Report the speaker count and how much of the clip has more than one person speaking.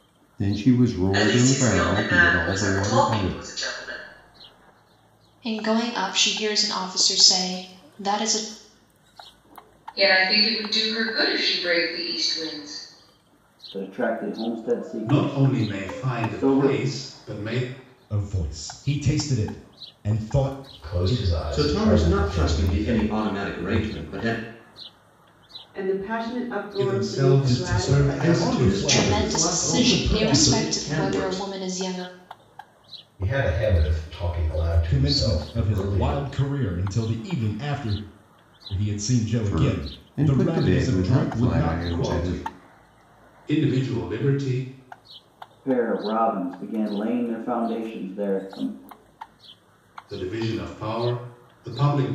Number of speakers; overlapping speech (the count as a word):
ten, about 31%